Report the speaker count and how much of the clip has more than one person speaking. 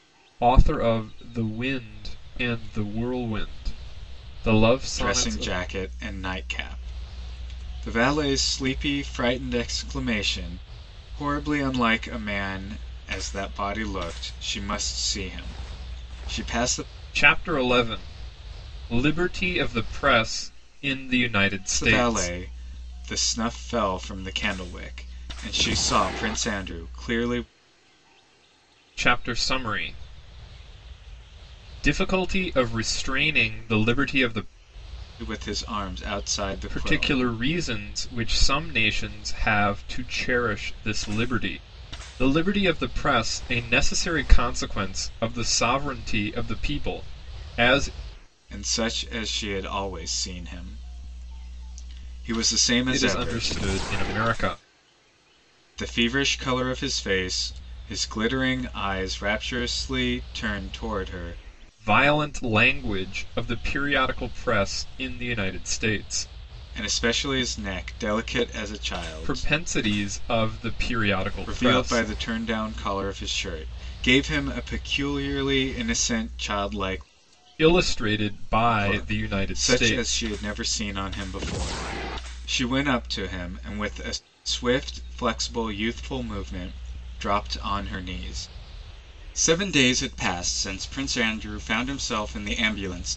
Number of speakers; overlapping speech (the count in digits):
2, about 6%